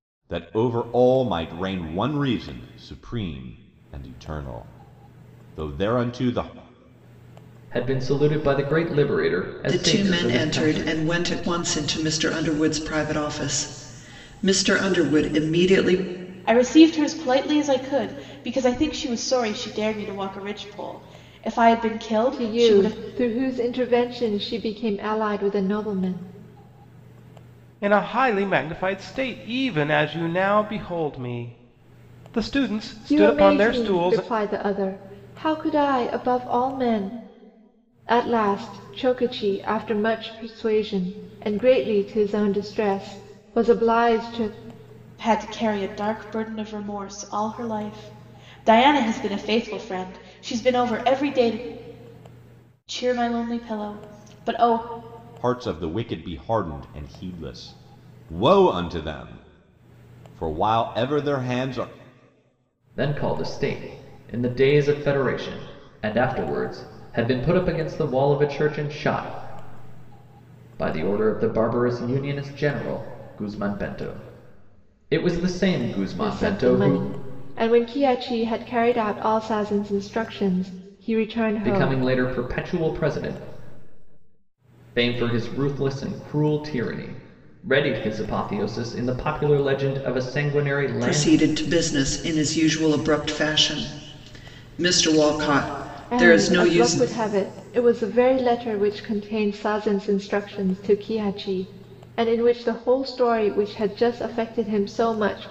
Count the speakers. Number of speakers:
6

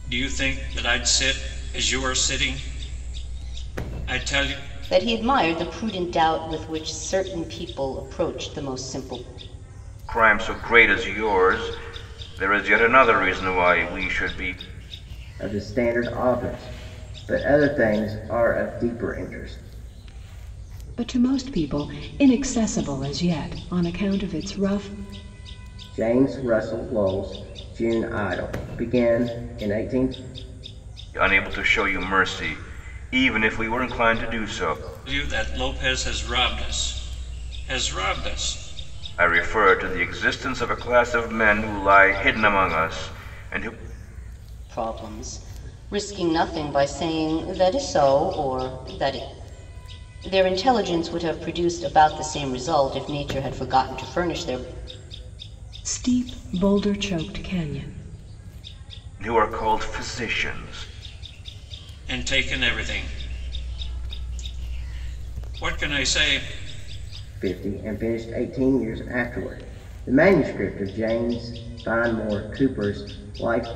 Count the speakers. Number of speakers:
5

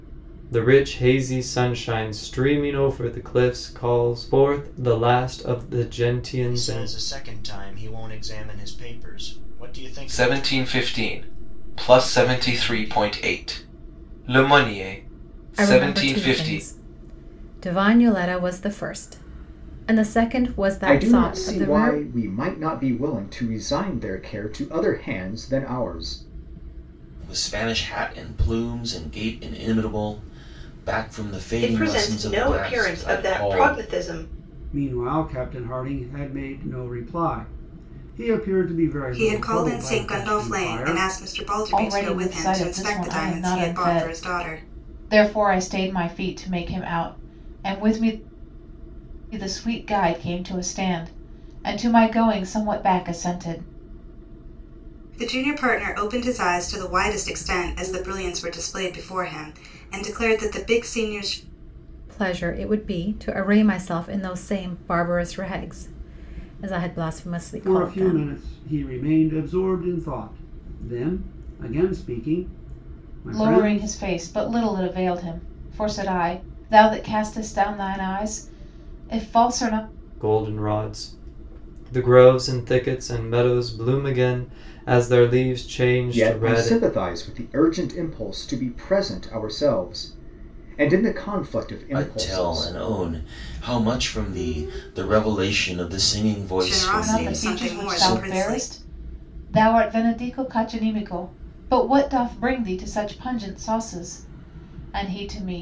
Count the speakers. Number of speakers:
10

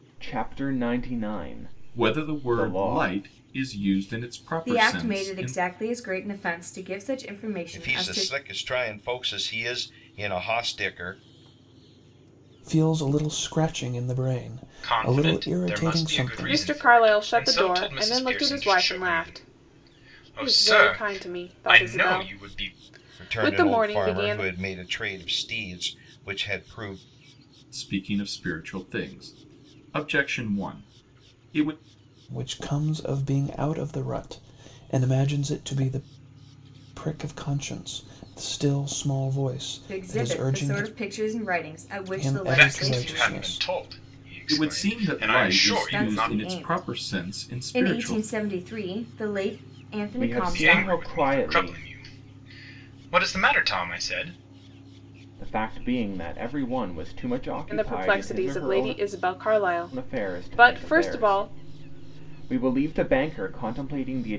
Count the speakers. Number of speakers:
7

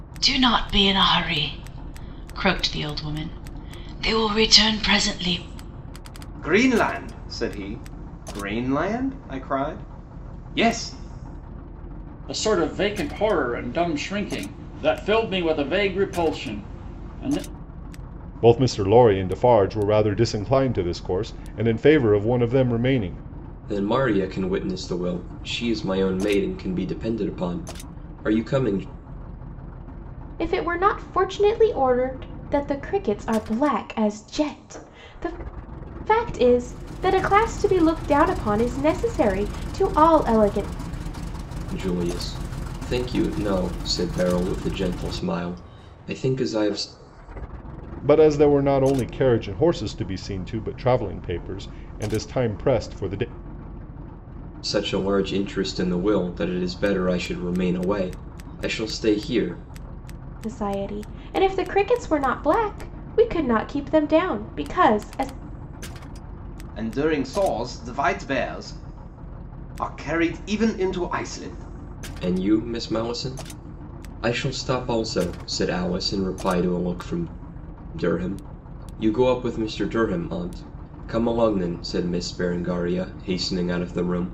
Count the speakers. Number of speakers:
6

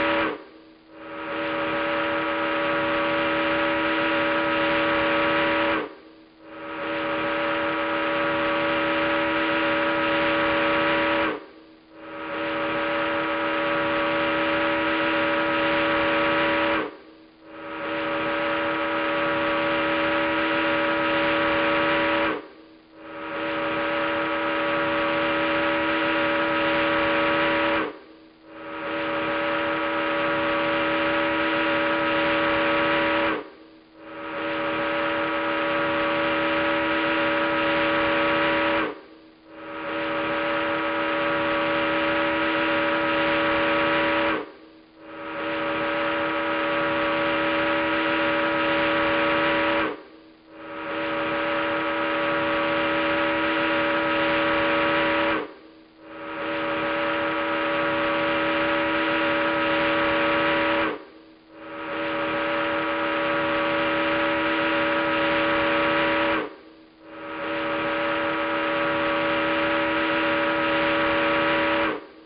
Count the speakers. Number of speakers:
0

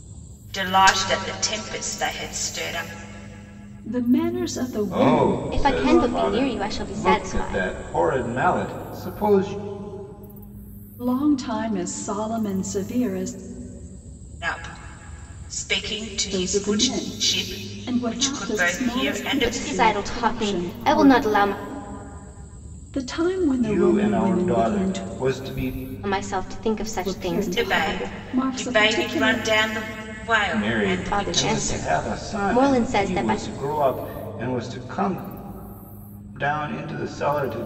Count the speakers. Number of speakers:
4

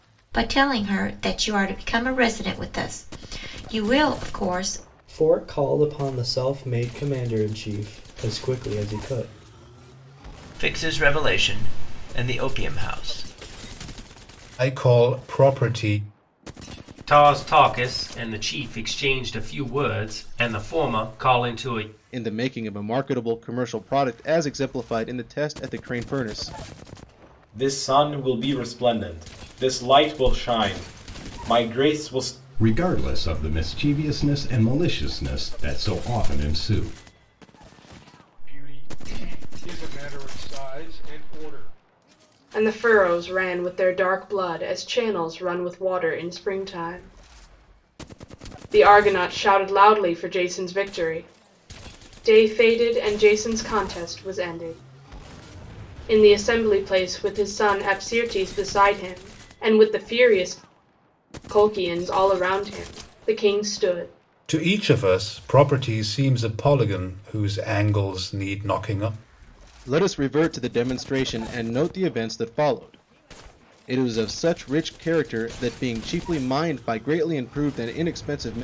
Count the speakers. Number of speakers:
10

